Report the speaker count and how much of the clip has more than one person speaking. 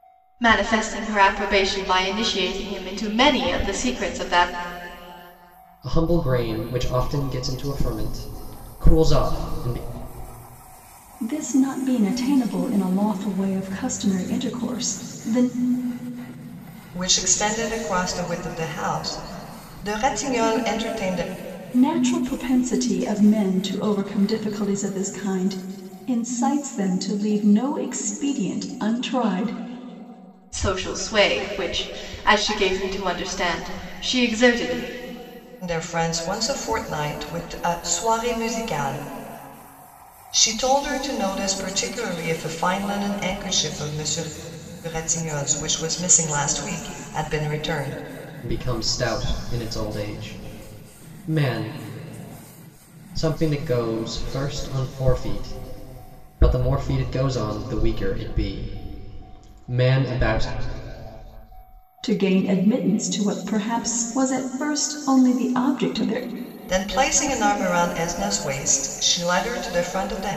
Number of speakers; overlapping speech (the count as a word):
four, no overlap